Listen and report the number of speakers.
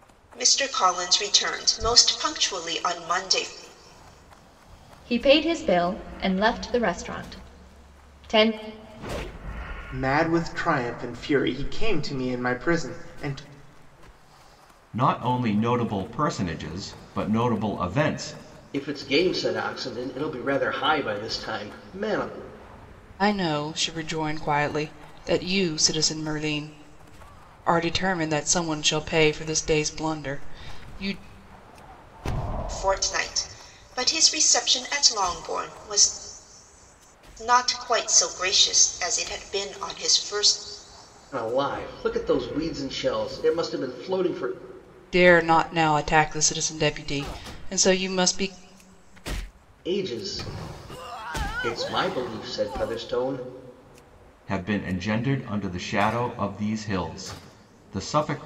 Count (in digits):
6